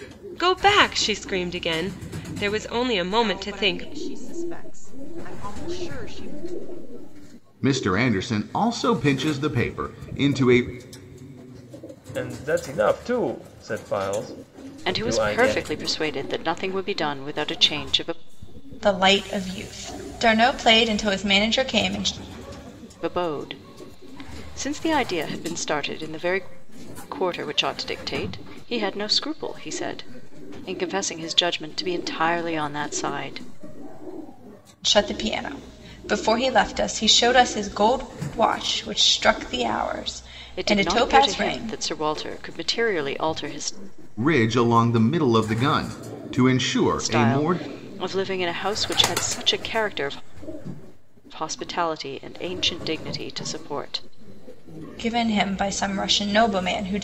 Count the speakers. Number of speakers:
6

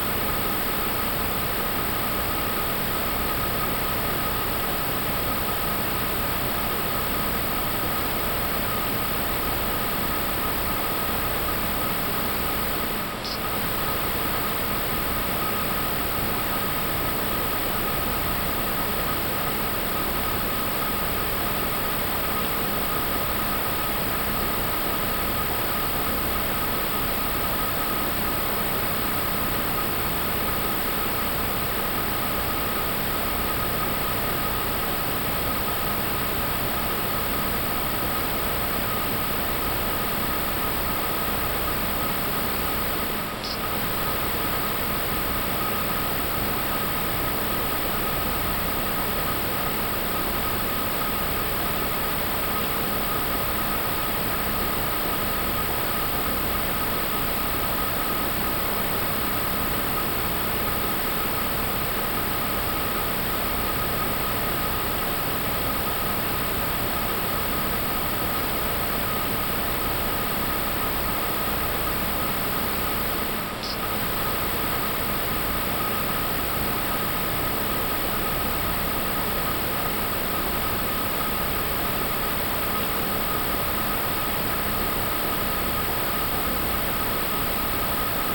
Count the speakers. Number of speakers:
0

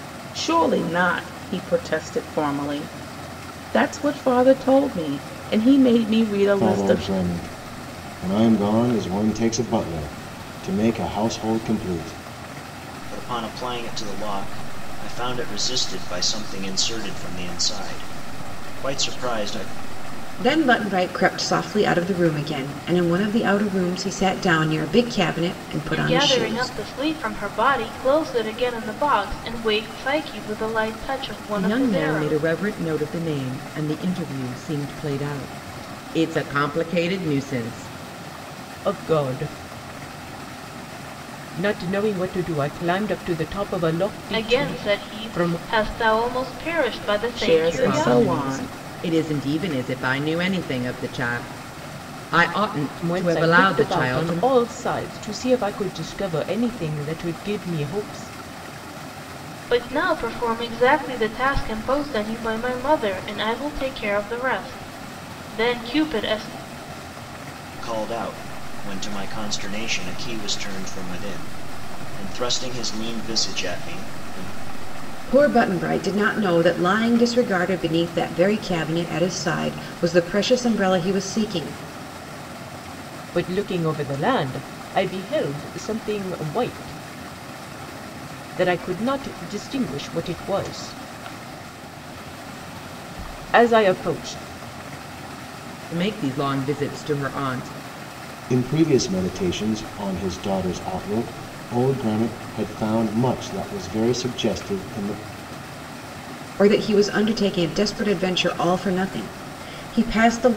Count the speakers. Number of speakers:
7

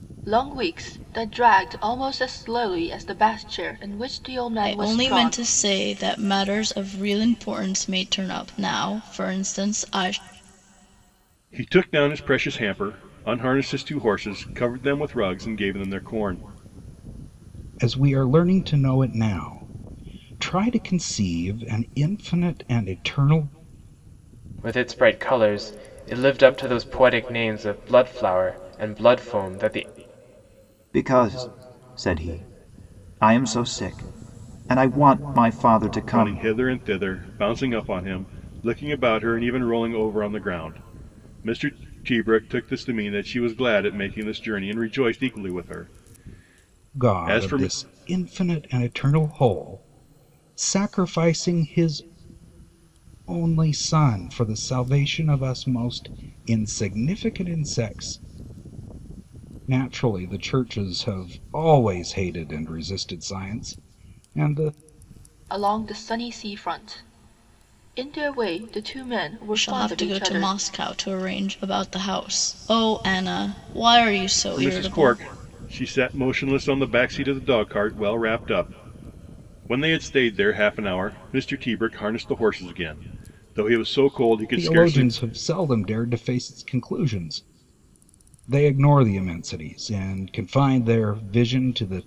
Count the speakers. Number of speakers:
6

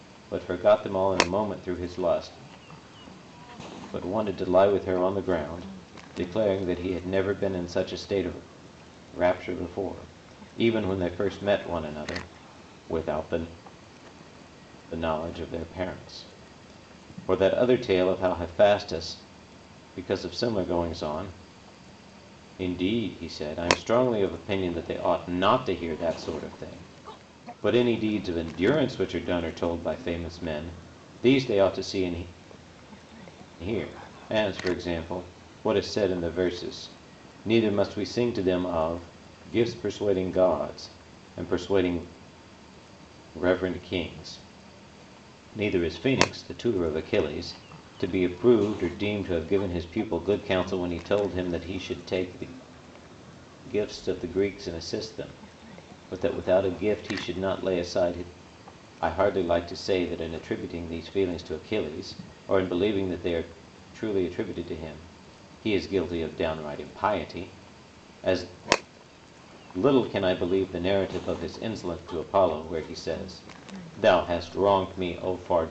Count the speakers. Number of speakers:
1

